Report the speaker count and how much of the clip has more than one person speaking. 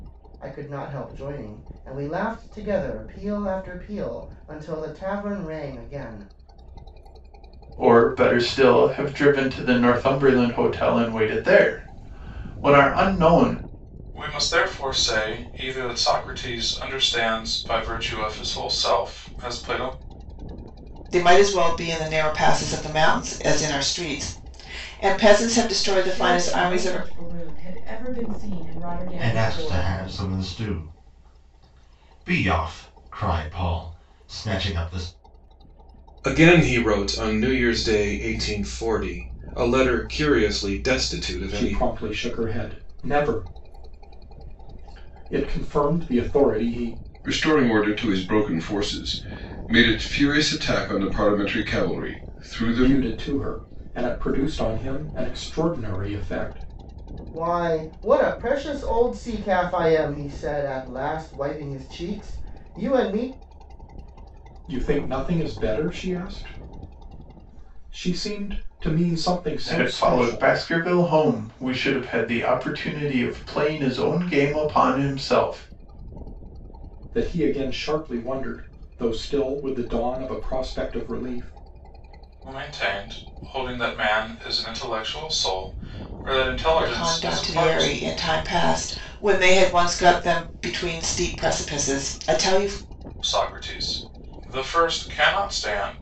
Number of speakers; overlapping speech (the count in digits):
9, about 5%